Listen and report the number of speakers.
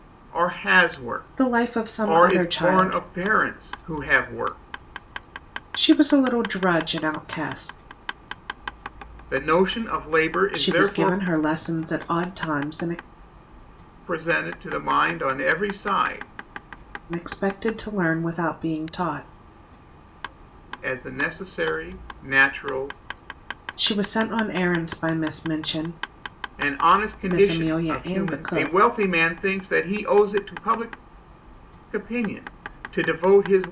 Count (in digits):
2